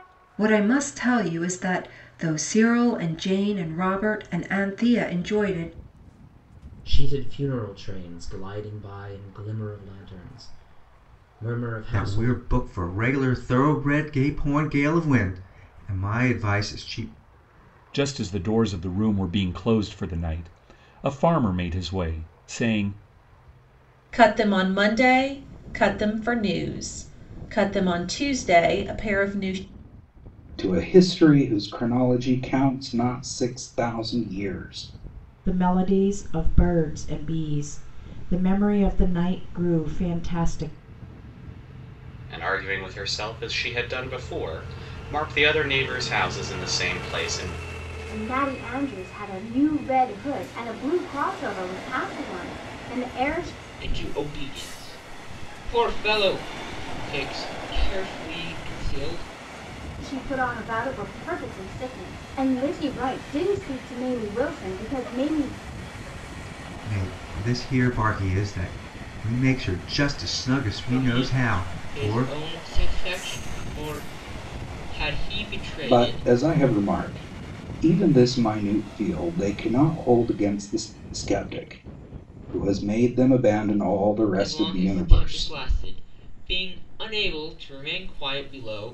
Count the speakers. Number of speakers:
ten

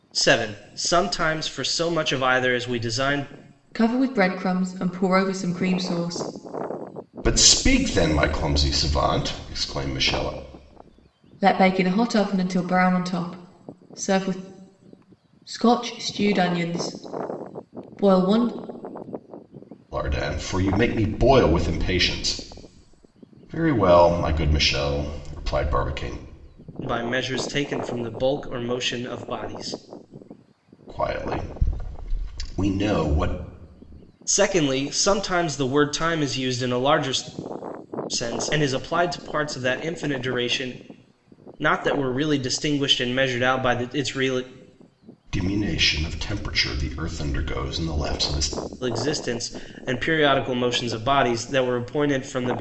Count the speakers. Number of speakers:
three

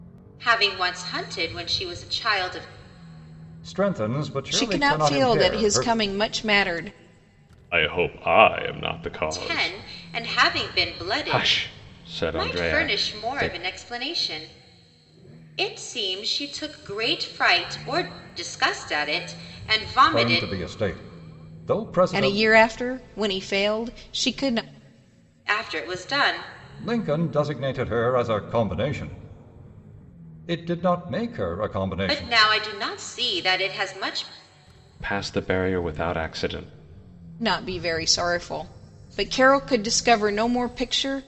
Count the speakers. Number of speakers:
four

